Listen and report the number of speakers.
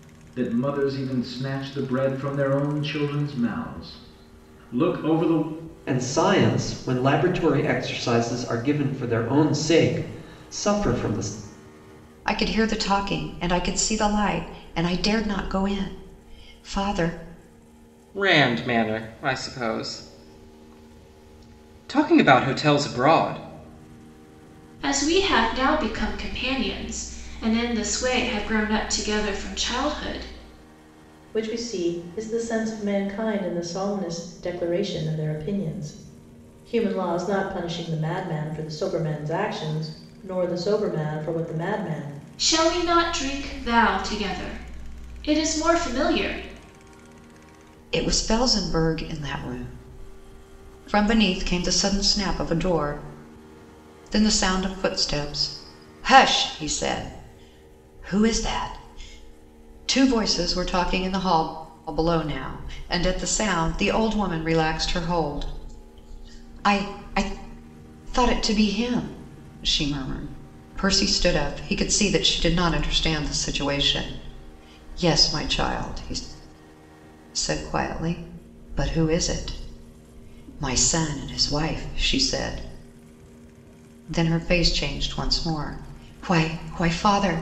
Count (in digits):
6